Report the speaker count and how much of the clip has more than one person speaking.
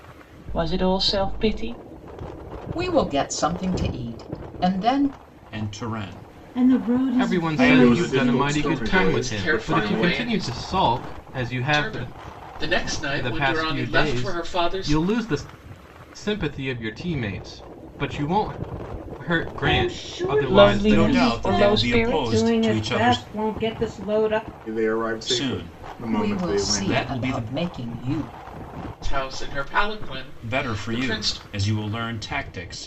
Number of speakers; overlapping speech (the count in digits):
7, about 40%